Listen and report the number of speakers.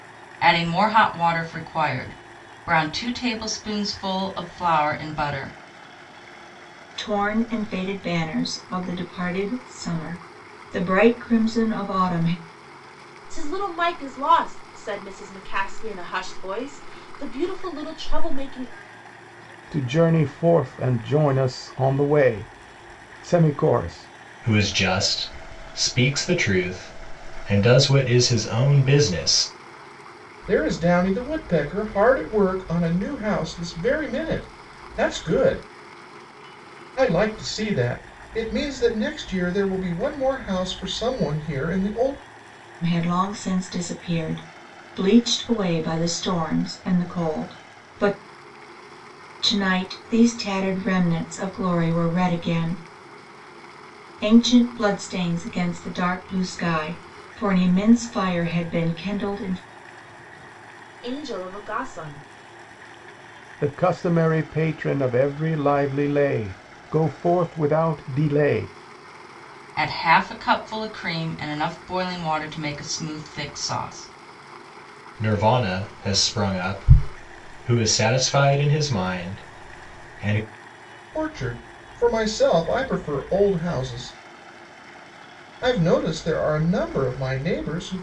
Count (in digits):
6